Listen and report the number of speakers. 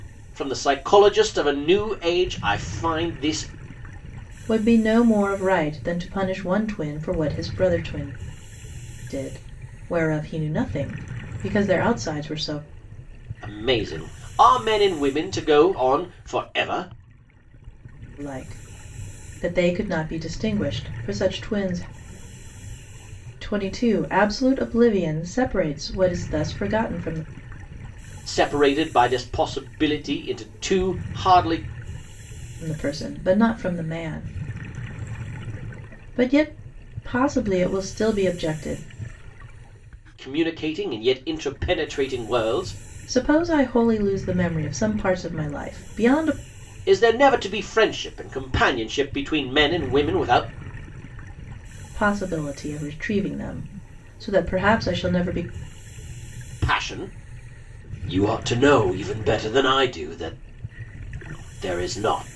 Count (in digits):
2